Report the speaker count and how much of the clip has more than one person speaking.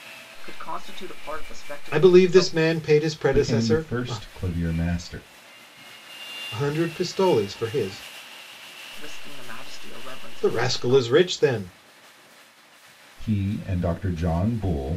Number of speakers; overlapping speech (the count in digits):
3, about 16%